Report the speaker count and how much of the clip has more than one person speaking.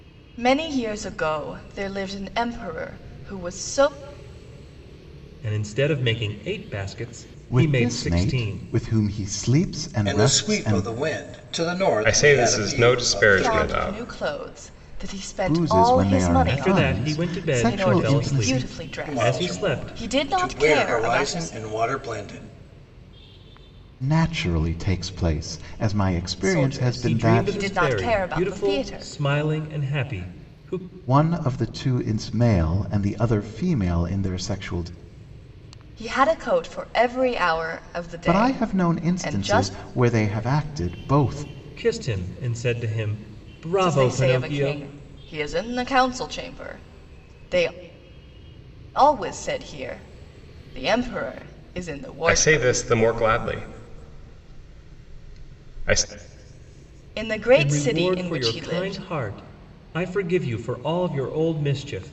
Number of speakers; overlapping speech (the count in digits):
5, about 28%